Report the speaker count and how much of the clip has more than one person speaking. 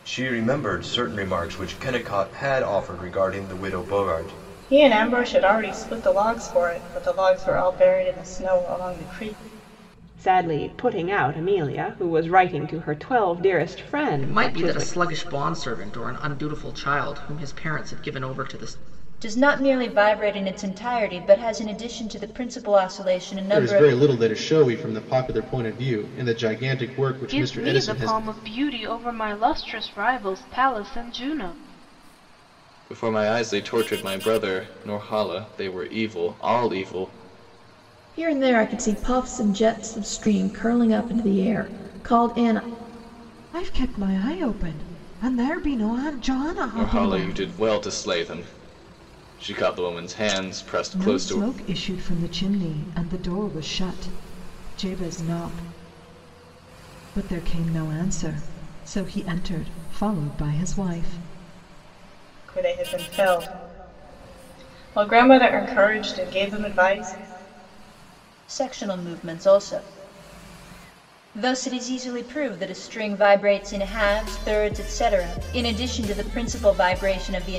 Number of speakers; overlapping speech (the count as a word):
ten, about 5%